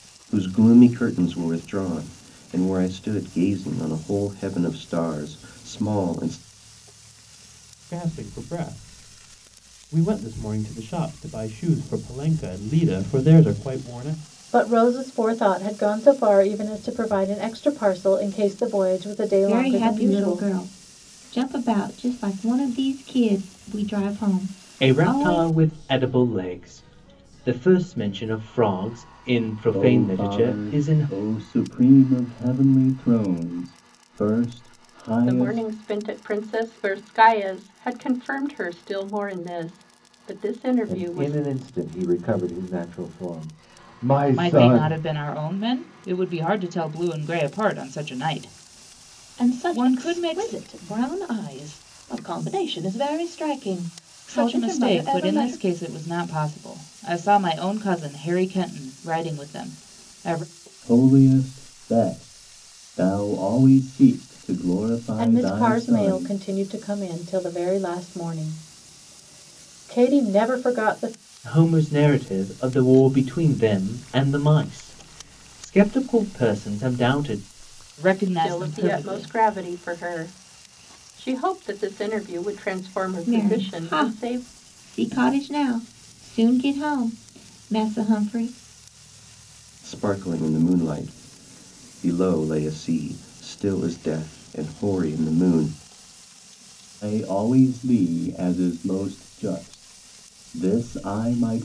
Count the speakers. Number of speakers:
ten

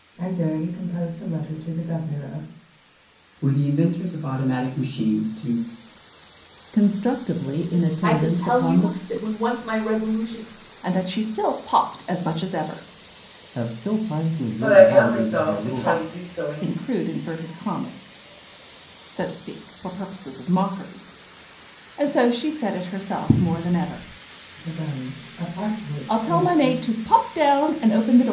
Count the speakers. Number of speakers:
seven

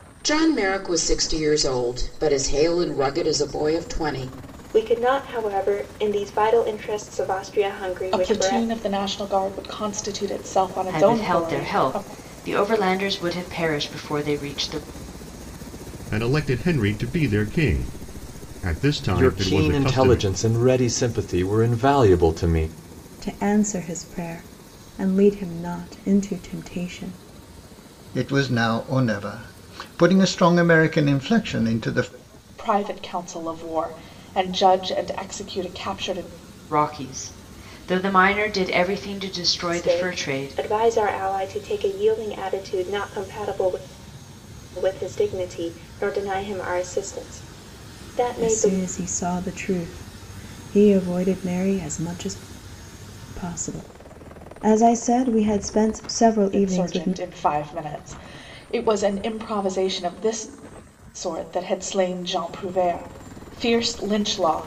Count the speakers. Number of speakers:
eight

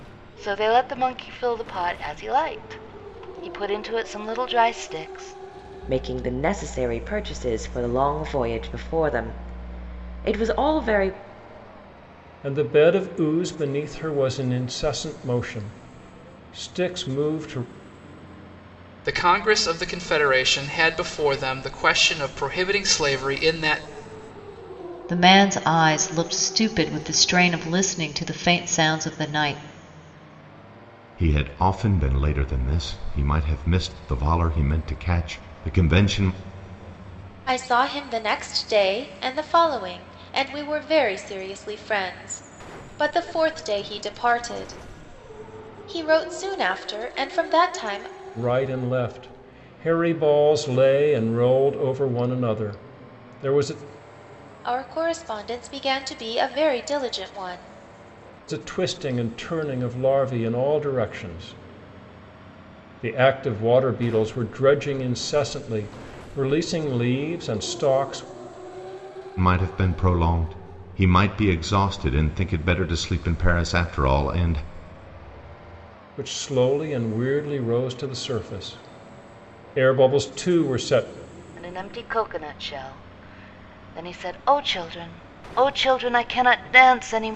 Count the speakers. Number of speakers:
seven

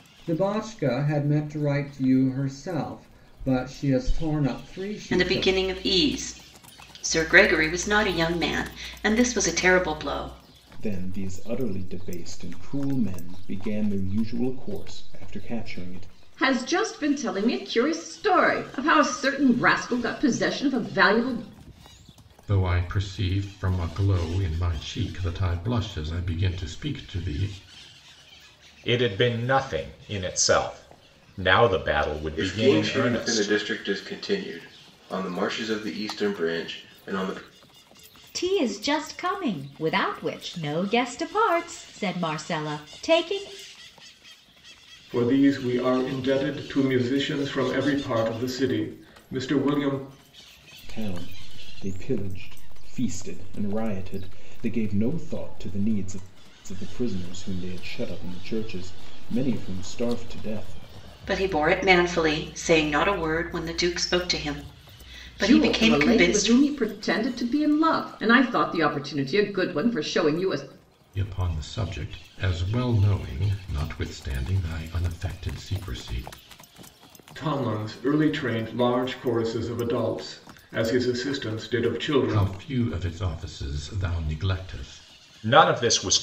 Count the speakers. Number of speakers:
nine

